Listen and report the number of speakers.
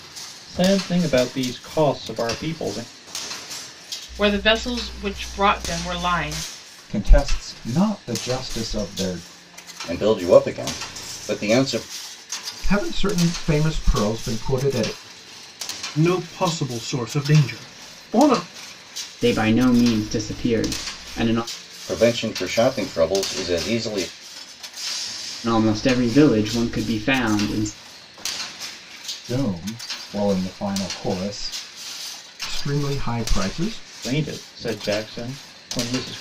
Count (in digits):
7